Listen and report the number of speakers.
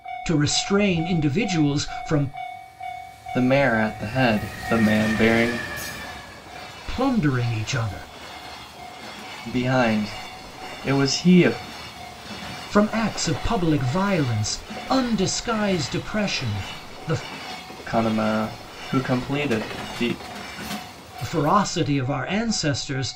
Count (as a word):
two